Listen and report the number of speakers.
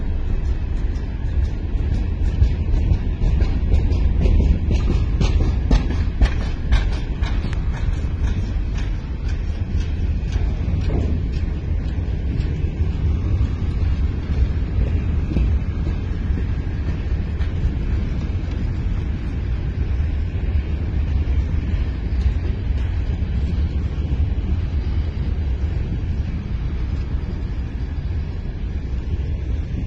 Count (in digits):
0